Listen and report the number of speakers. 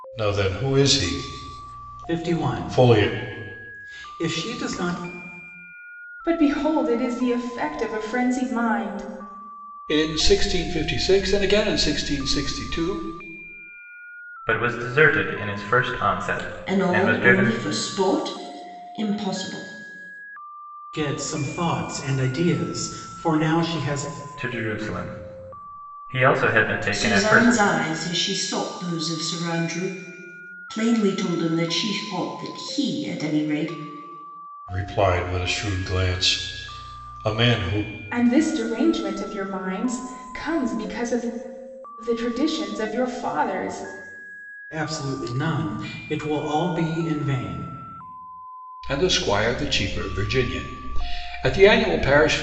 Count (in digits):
6